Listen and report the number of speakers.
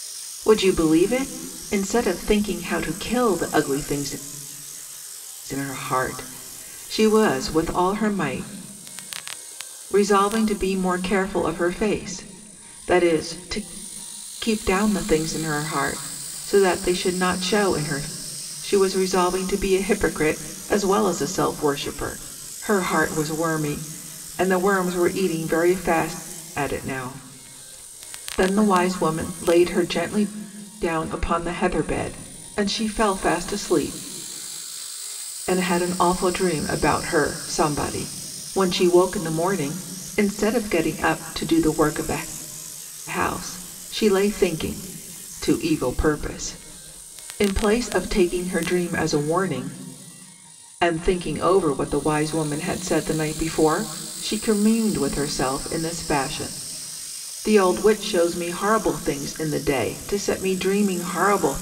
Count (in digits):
1